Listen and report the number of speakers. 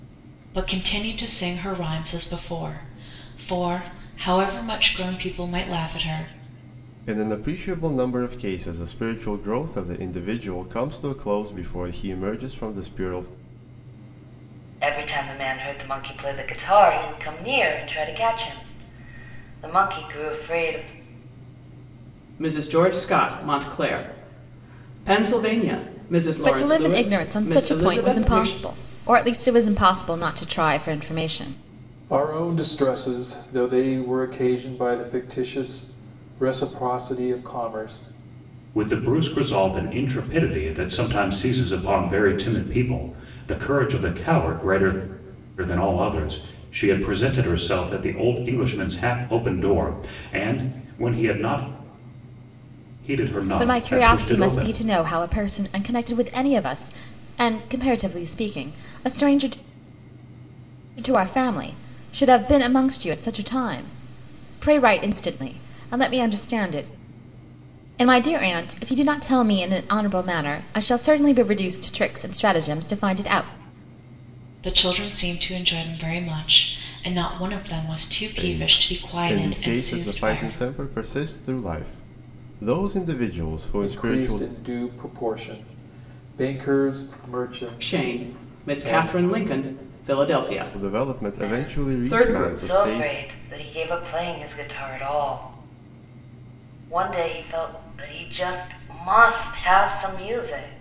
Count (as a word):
seven